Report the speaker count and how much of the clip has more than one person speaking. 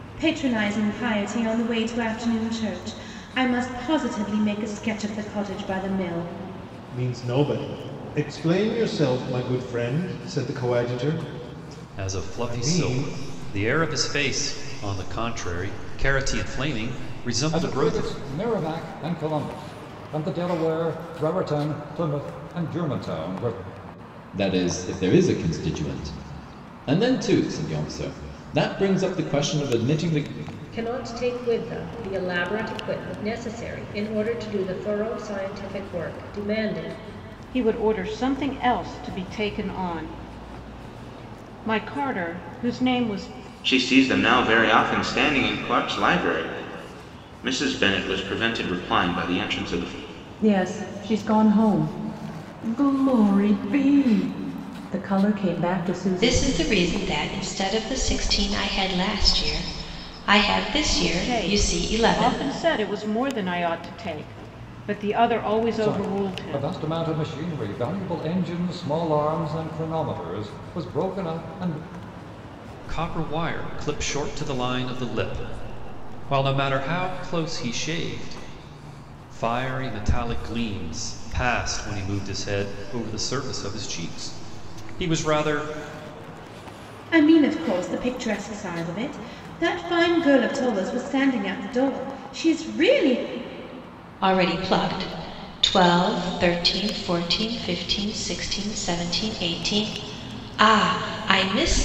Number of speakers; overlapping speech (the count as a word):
ten, about 4%